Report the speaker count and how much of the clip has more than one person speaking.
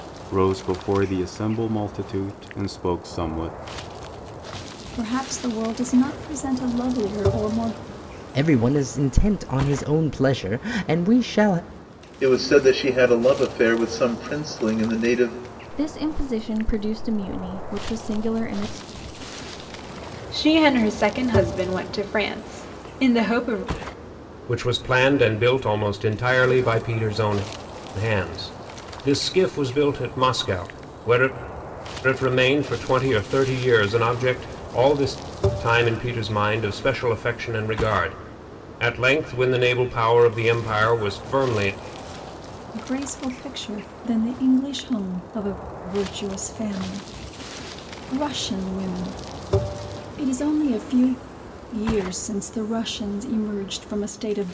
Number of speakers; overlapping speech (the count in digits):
7, no overlap